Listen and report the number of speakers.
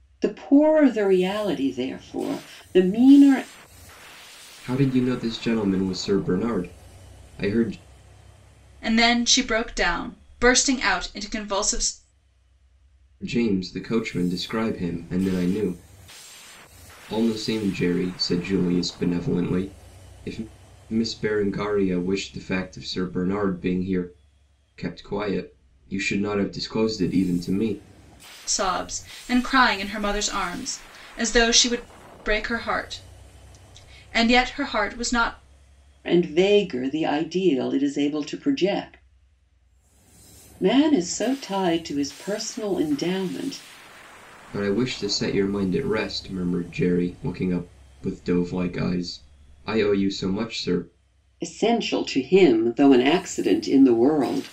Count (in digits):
3